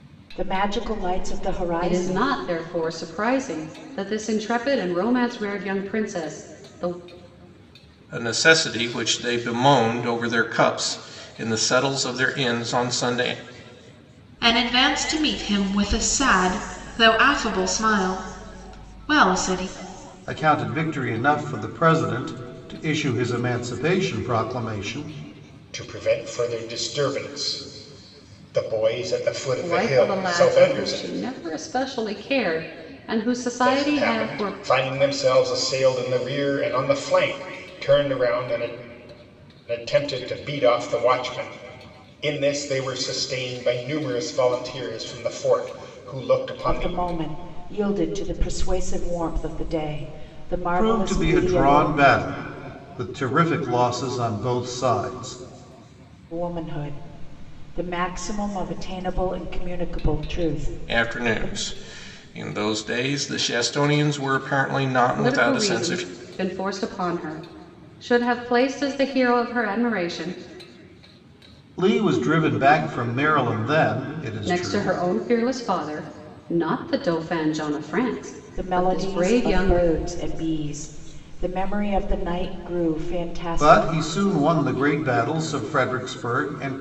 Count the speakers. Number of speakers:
6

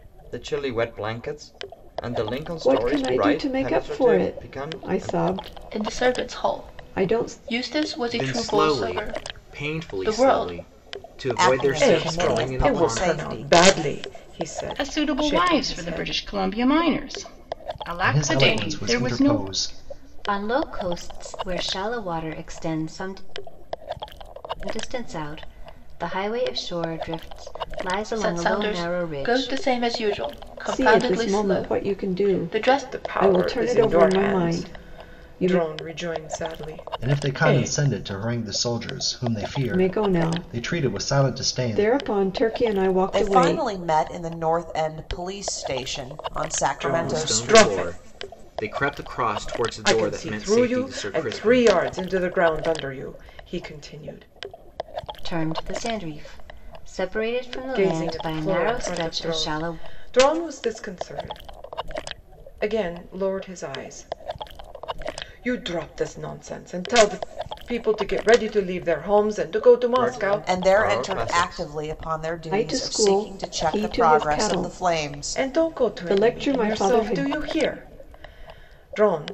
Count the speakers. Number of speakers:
9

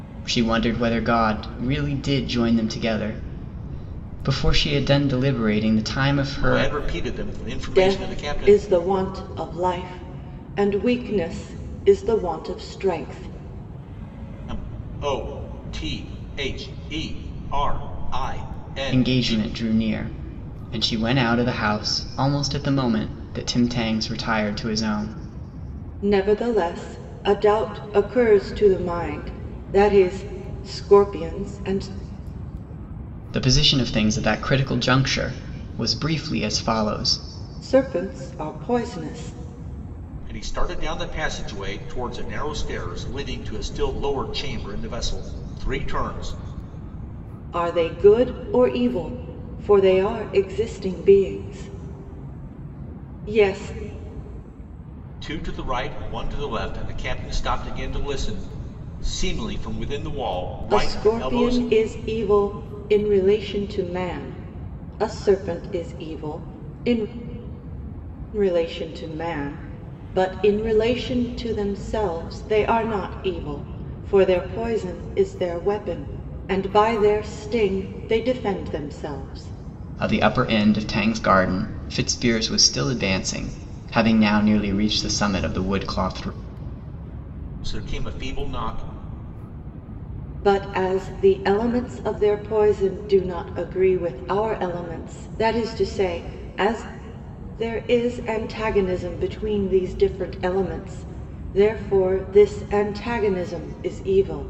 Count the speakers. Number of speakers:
3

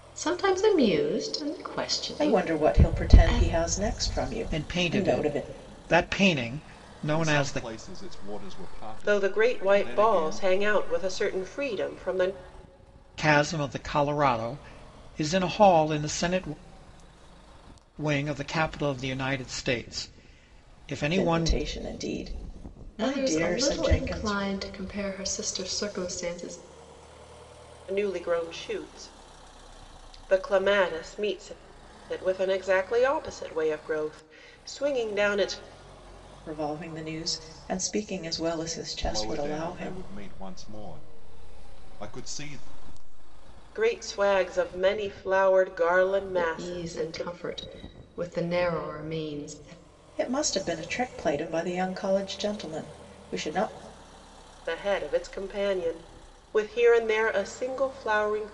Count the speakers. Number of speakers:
5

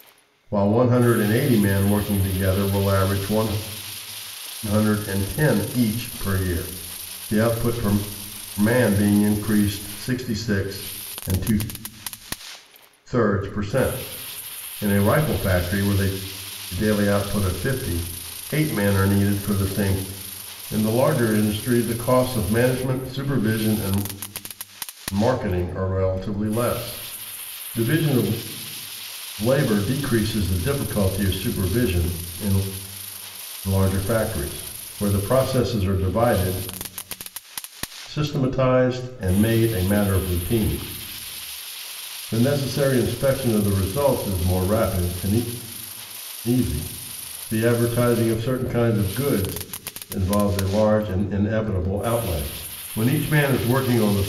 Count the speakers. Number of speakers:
1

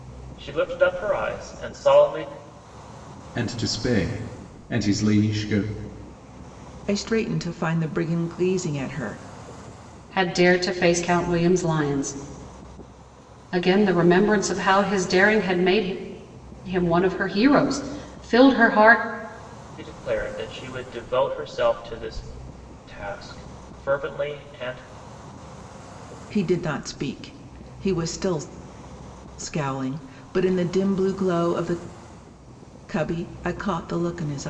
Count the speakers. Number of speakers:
4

